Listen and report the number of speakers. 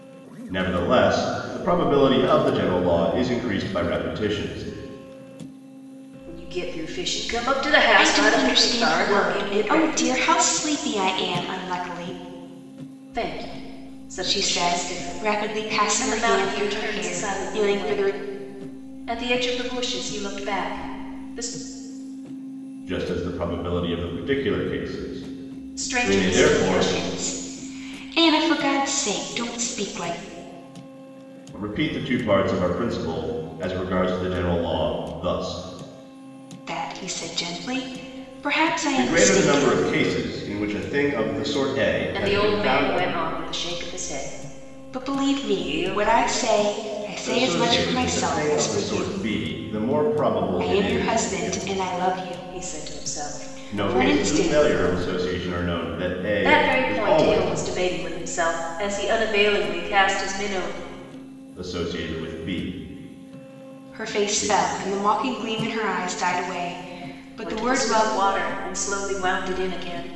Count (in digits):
3